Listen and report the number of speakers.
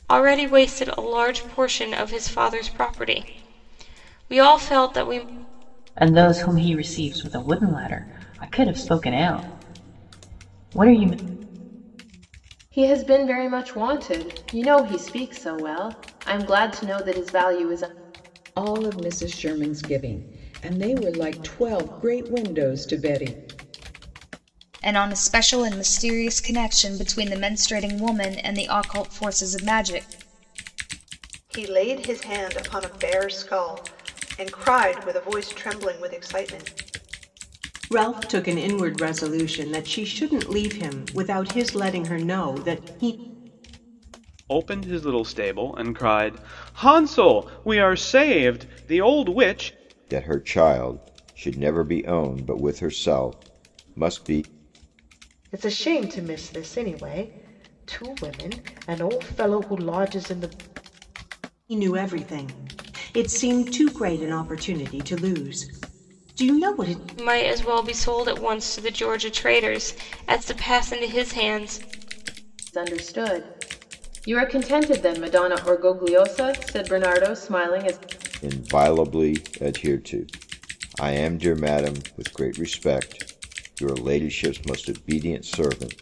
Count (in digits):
10